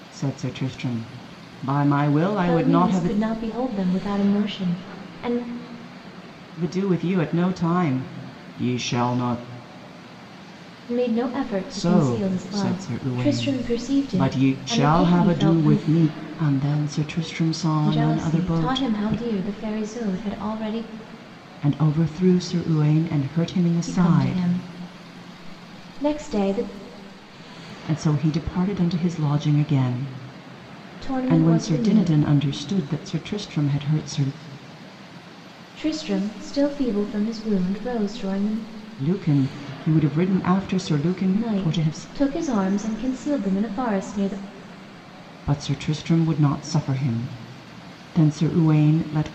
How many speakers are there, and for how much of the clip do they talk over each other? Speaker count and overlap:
2, about 17%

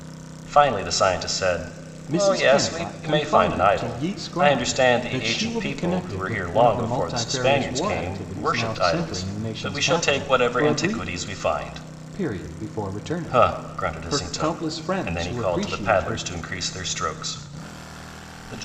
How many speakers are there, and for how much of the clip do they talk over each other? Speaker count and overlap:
2, about 60%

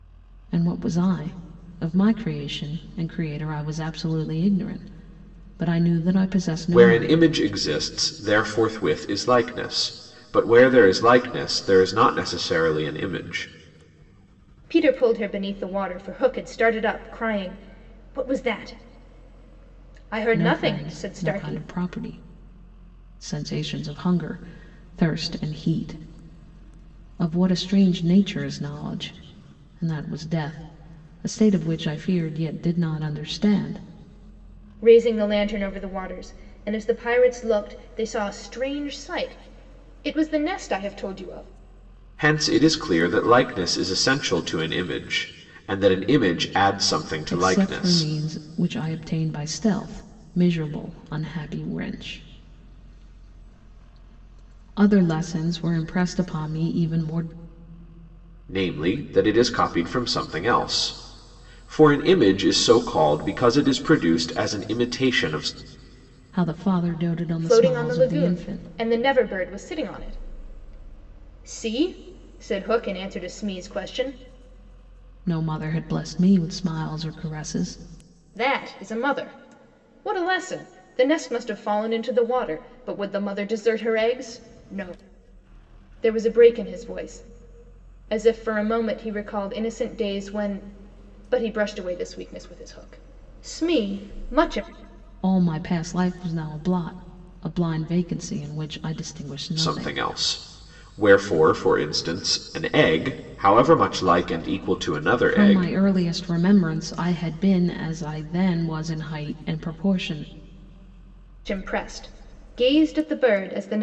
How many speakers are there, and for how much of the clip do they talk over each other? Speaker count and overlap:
3, about 4%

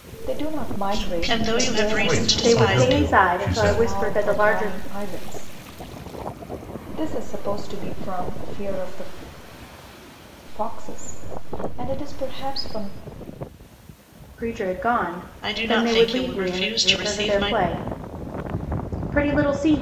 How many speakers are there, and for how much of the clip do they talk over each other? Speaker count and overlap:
5, about 30%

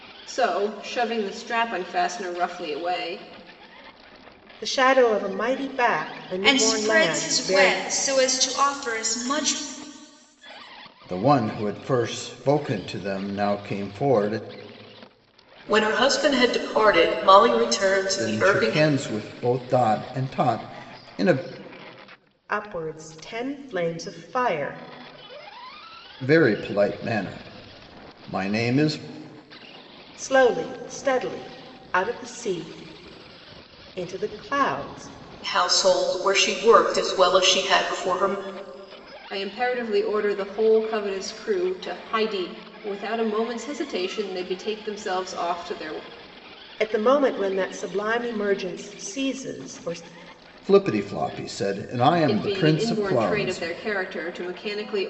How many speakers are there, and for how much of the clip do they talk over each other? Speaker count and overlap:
5, about 6%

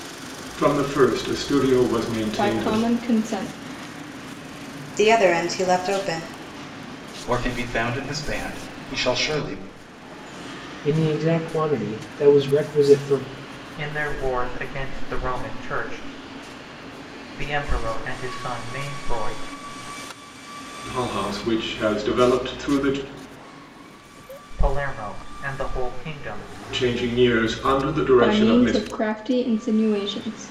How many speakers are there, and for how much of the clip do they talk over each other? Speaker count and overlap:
6, about 4%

